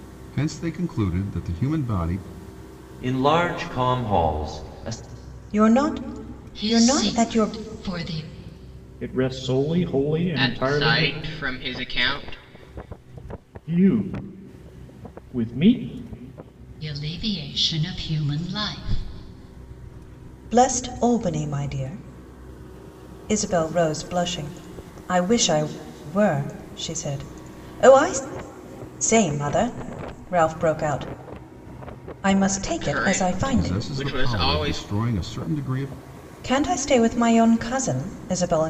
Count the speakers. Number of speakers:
6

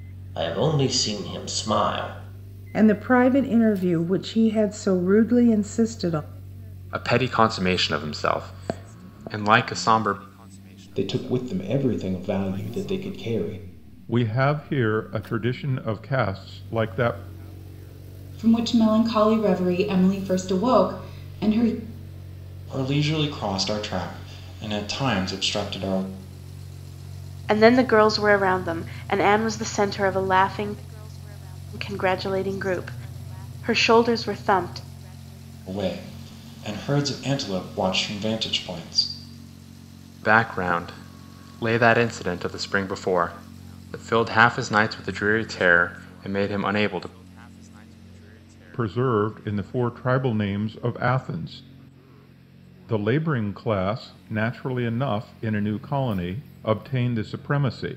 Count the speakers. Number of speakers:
8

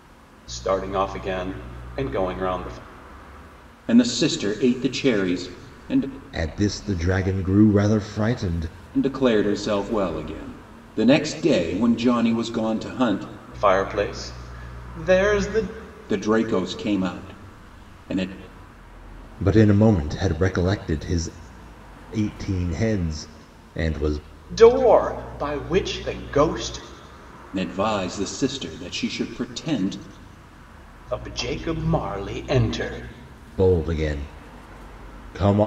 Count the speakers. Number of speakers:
3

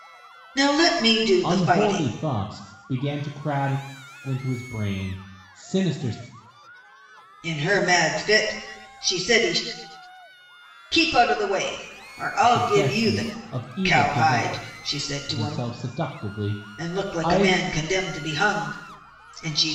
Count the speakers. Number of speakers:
2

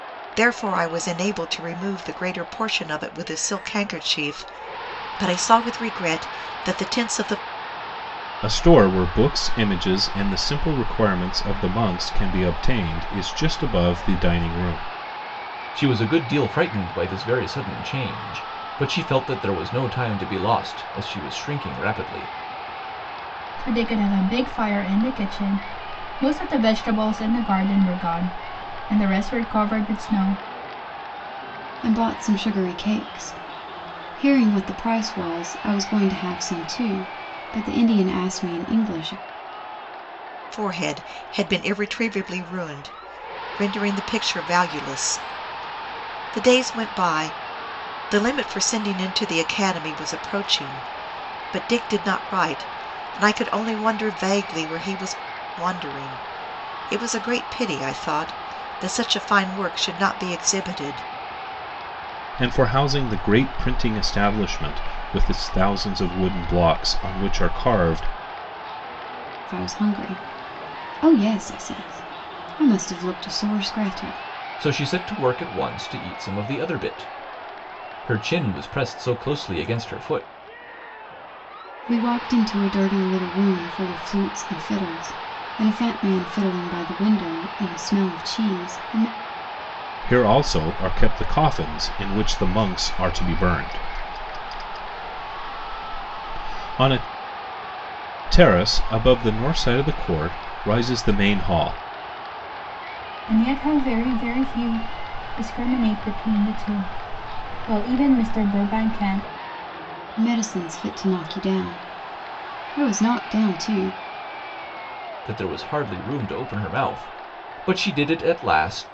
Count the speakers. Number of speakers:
5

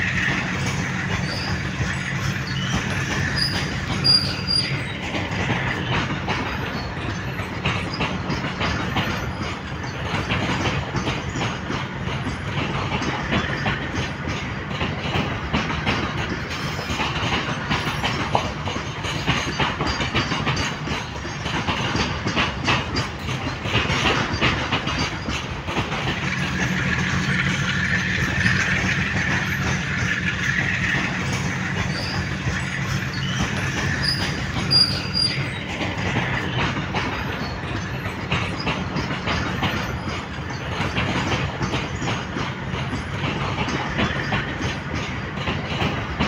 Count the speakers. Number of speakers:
0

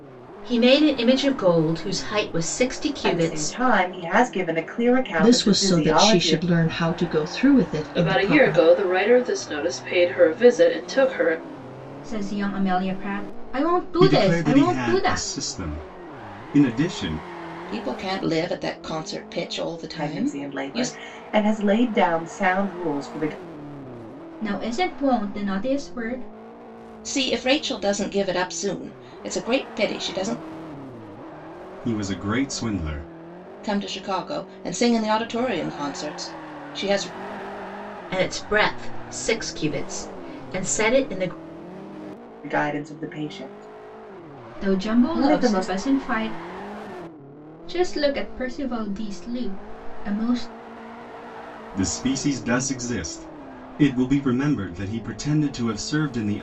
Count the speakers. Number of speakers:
7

